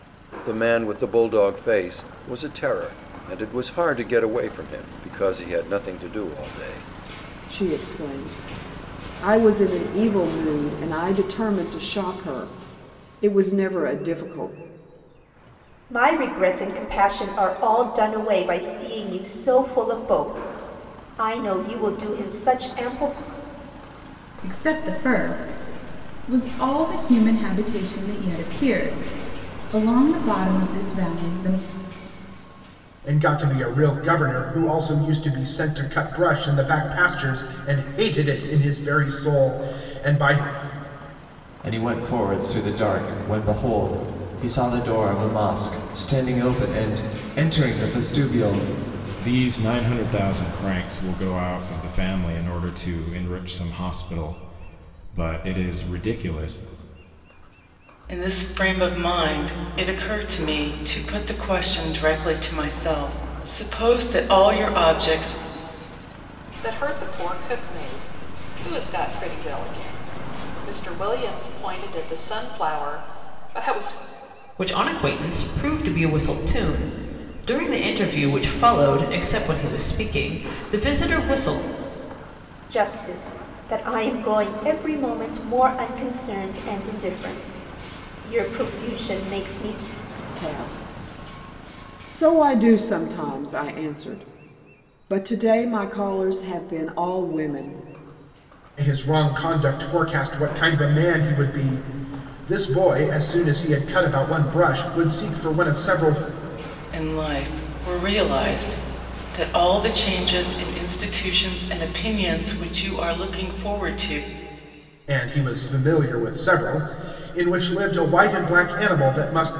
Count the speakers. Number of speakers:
10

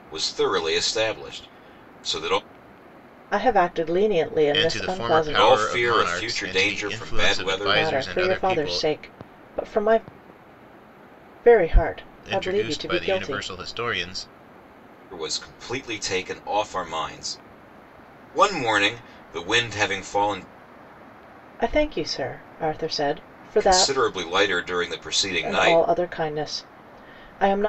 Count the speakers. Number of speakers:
3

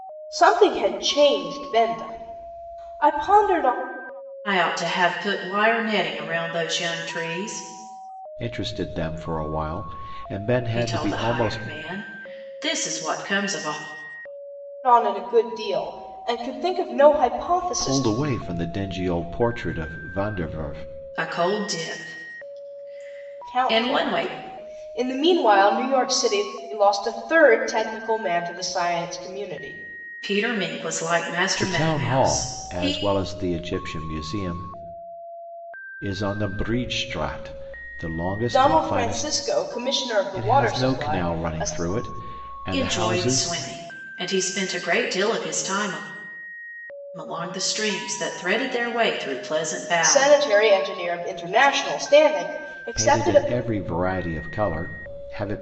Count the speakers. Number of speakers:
3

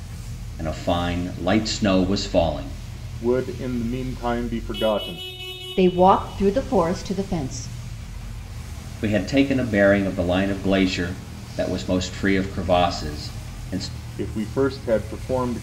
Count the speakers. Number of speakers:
3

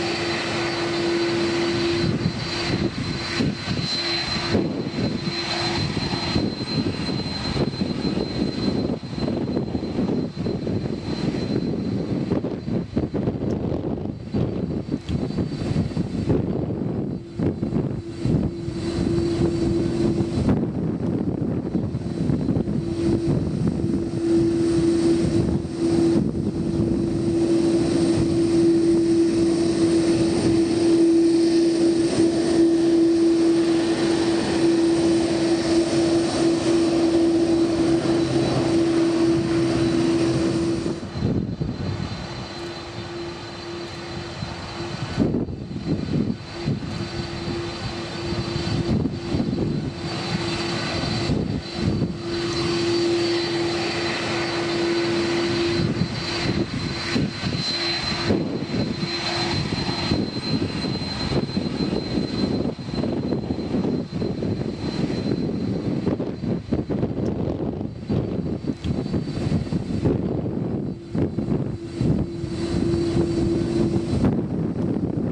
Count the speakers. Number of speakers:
0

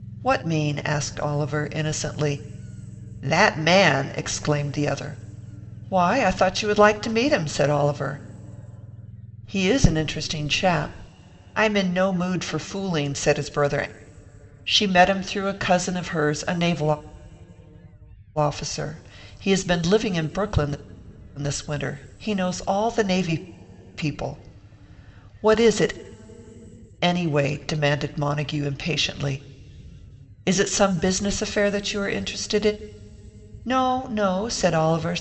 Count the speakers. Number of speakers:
1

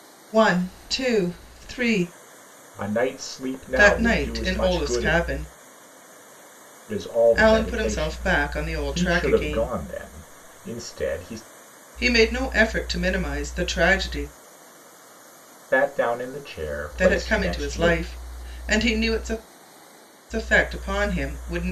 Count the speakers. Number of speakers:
2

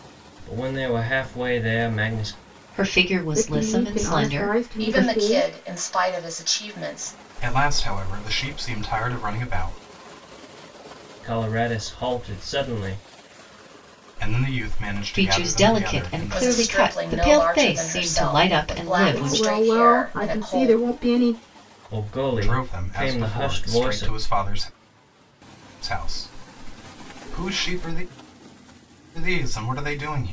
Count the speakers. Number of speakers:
5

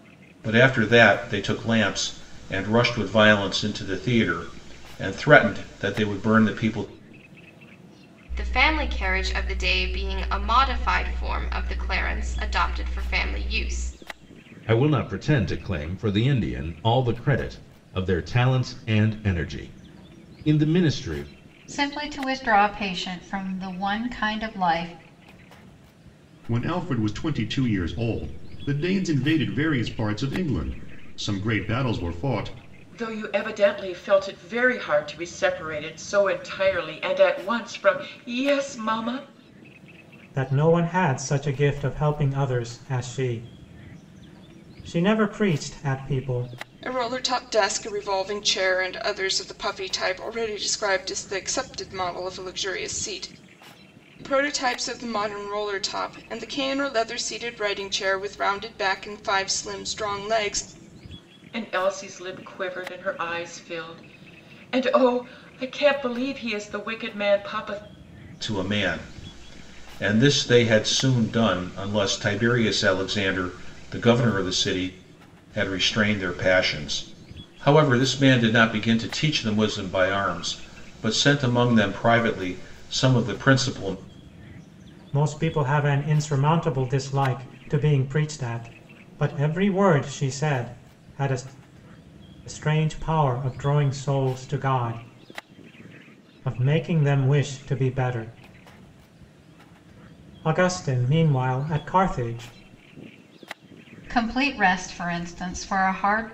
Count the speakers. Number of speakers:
8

